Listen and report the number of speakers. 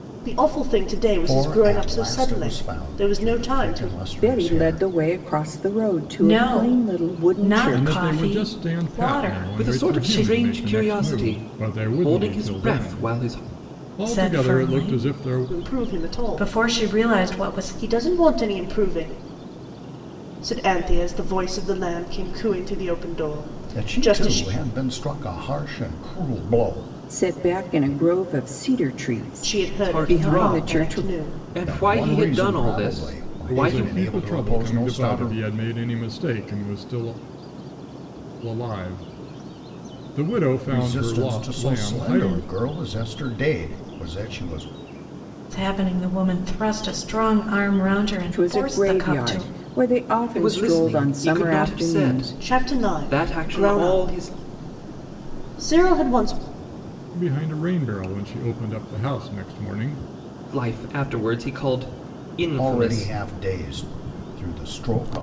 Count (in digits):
6